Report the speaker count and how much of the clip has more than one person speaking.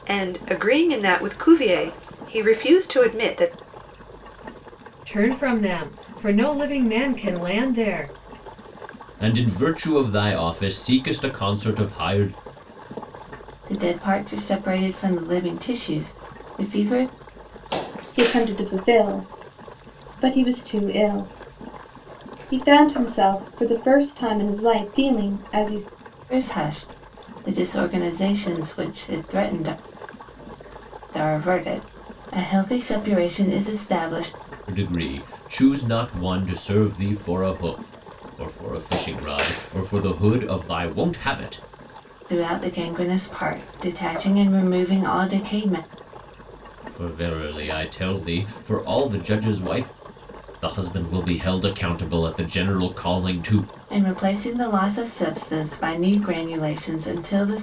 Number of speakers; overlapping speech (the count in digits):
5, no overlap